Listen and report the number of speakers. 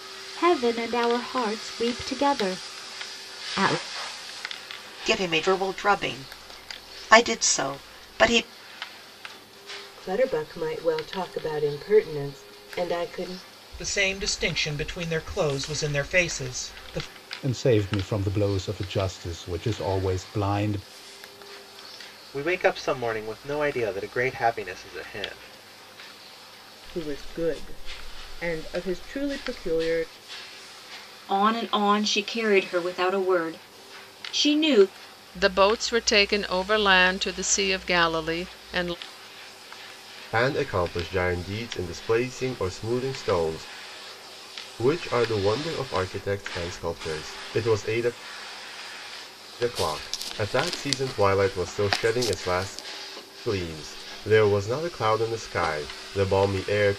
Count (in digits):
10